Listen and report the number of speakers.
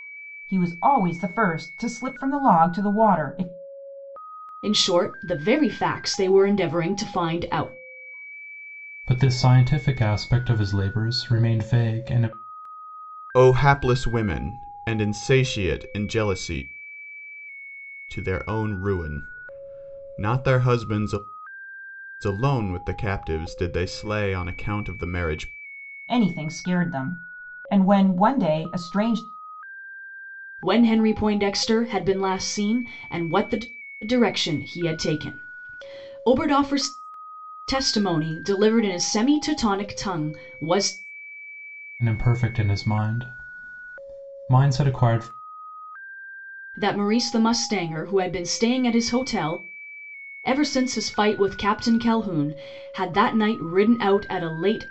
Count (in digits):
4